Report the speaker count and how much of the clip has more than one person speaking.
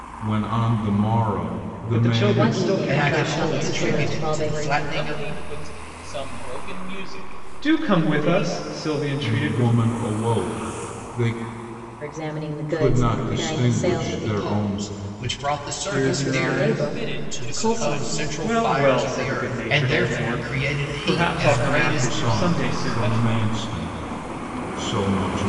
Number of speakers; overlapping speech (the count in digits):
5, about 57%